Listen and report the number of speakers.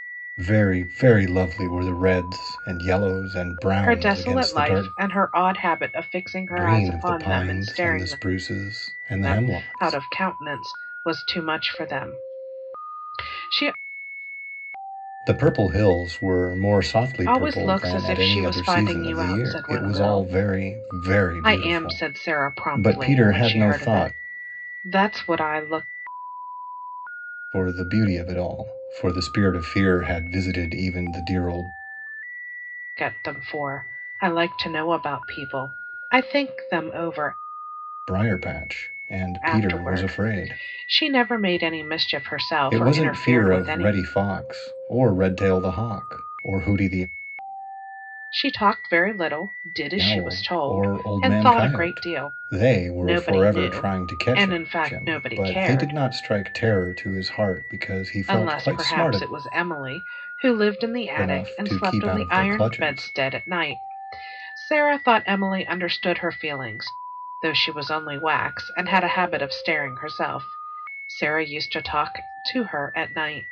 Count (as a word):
two